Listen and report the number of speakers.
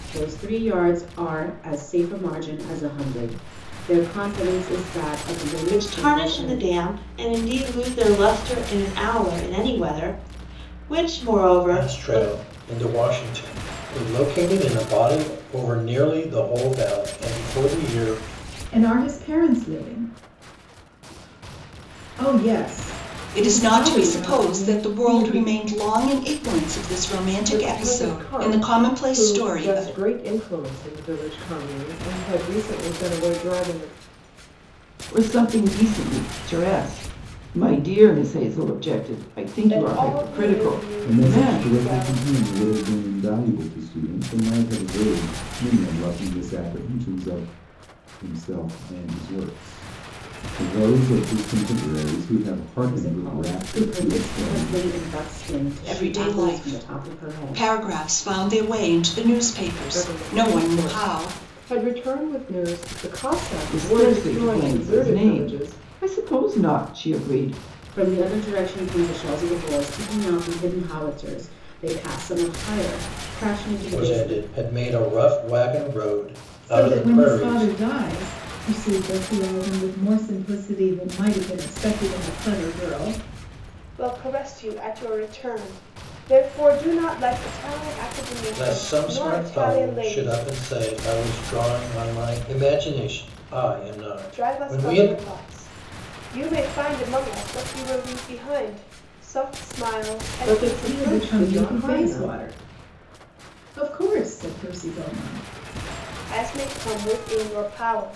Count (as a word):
nine